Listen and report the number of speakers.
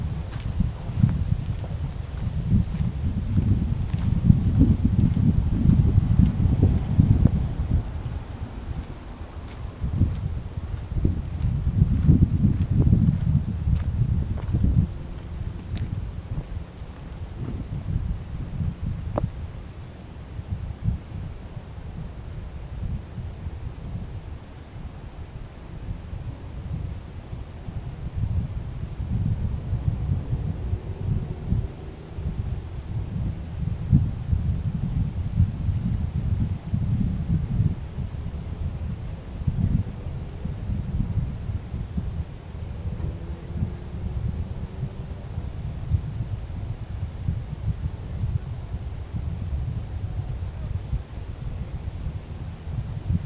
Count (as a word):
zero